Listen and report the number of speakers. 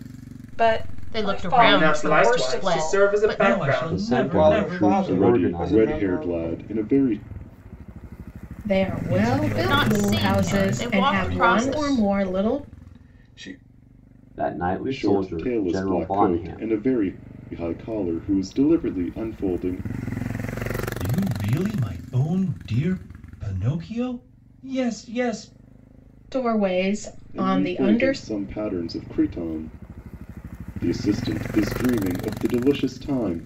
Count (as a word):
eight